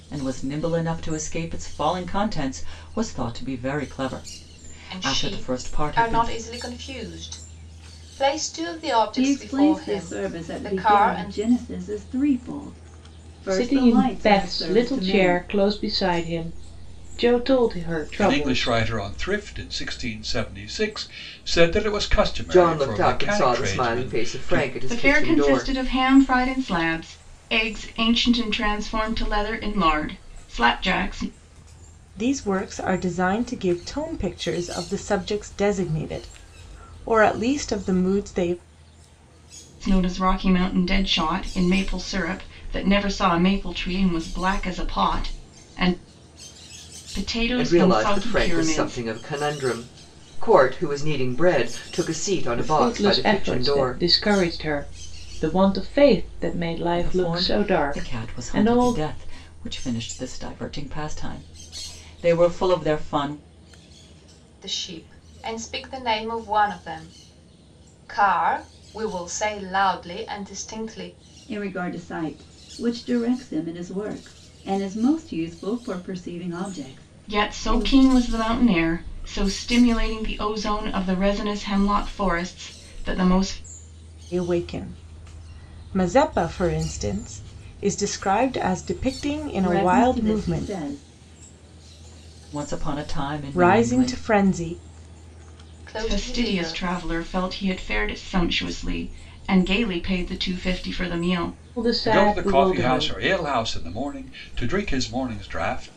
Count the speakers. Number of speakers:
eight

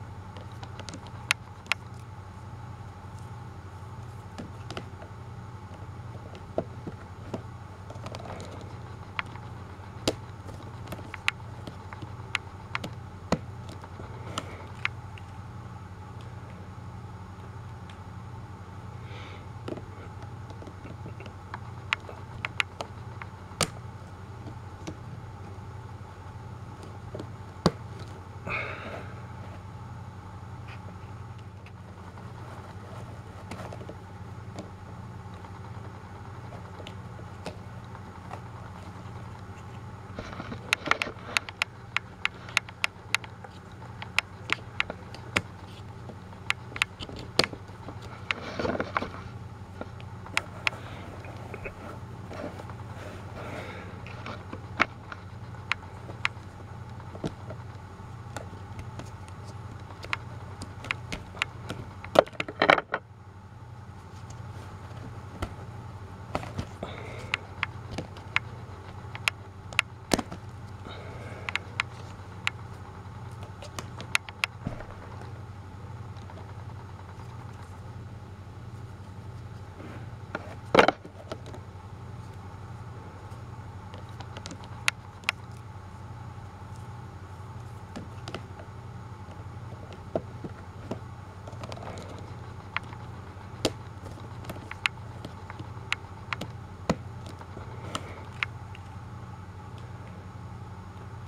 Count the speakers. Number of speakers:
zero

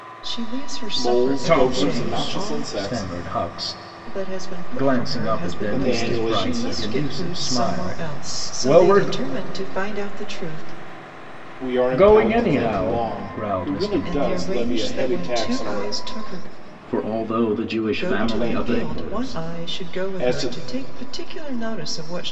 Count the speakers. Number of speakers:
three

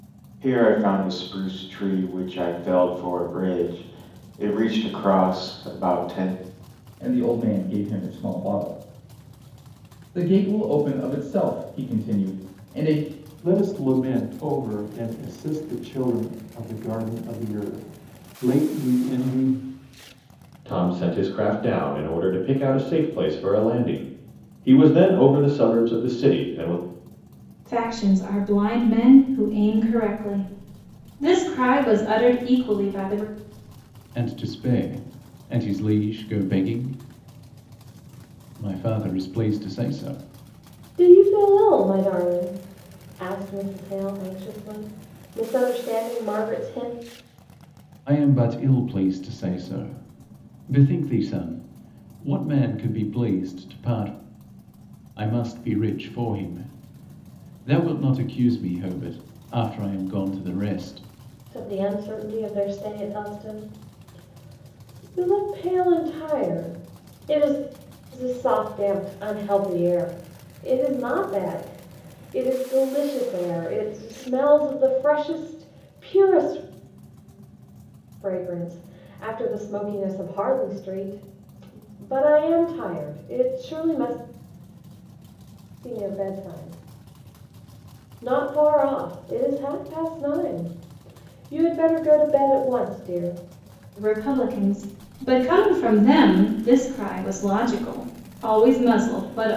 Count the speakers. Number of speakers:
seven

